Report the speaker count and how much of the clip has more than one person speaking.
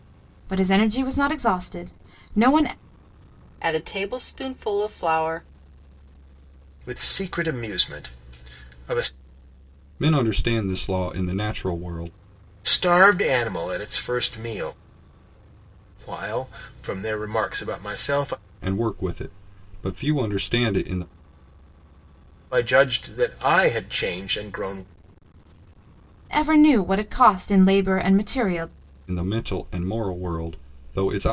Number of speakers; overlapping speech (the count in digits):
4, no overlap